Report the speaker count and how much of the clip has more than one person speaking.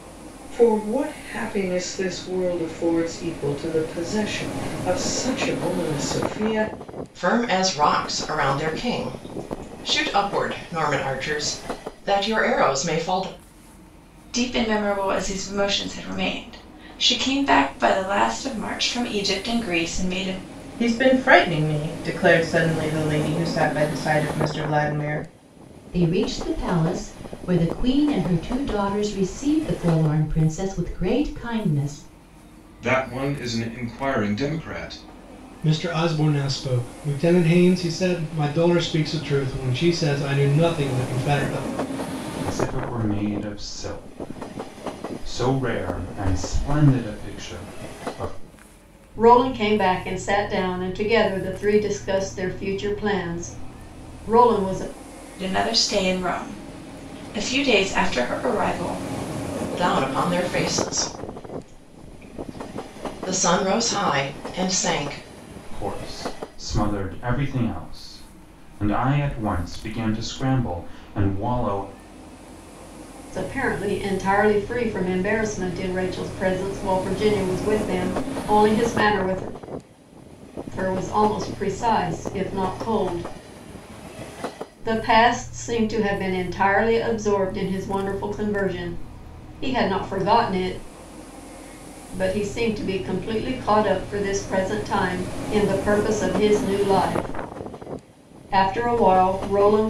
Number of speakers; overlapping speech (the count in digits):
9, no overlap